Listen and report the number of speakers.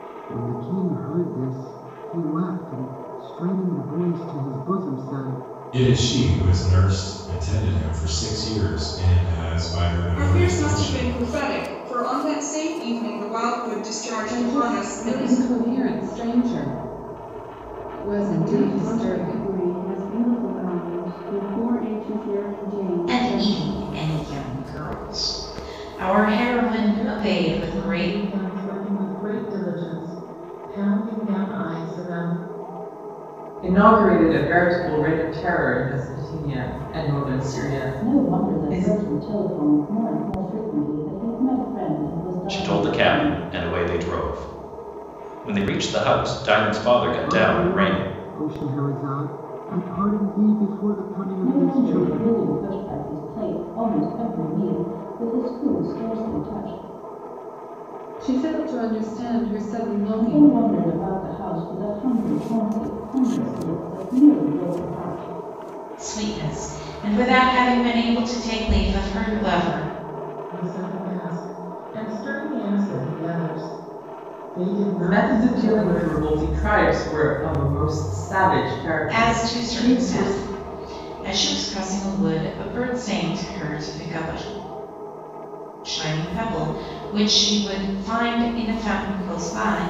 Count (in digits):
10